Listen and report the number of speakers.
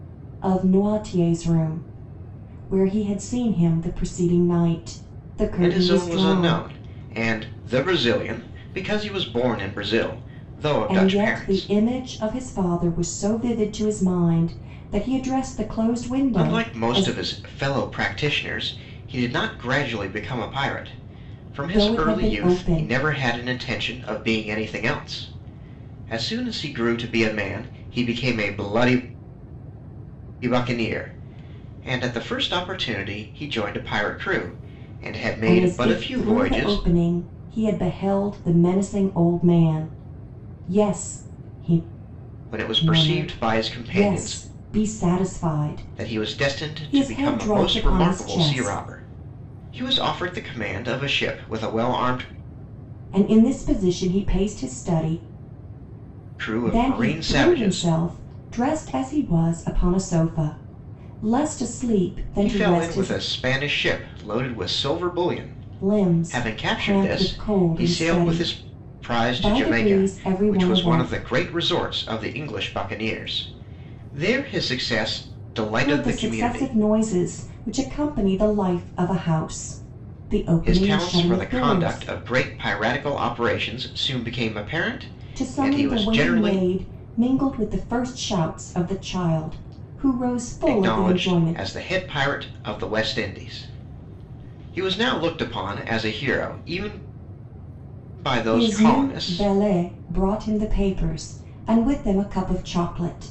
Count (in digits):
2